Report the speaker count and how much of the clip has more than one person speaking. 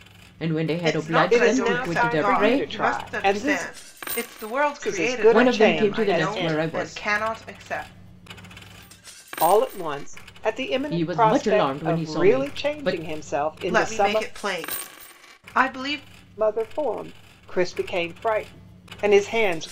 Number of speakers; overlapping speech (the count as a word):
three, about 40%